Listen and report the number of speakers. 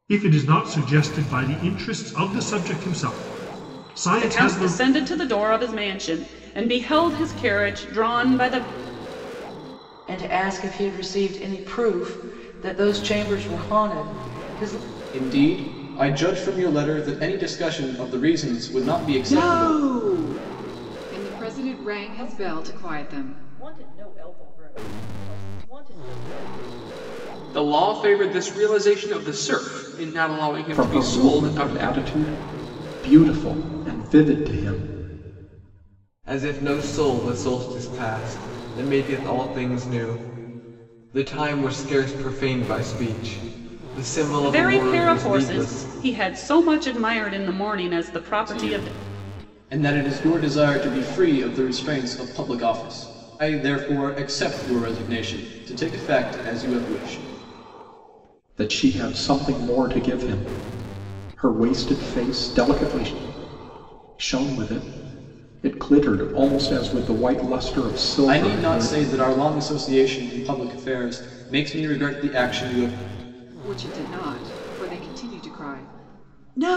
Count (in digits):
9